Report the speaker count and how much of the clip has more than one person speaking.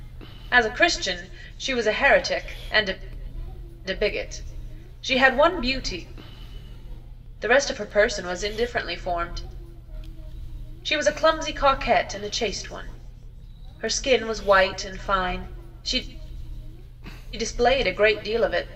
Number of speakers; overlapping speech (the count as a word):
one, no overlap